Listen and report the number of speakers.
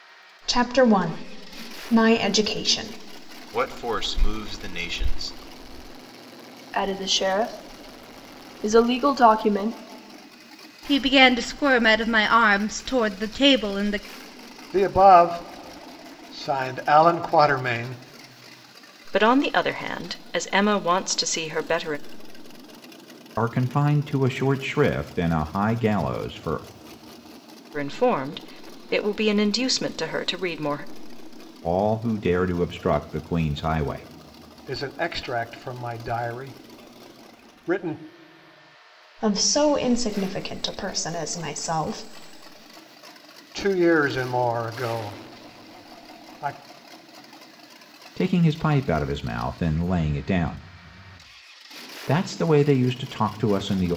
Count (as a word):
seven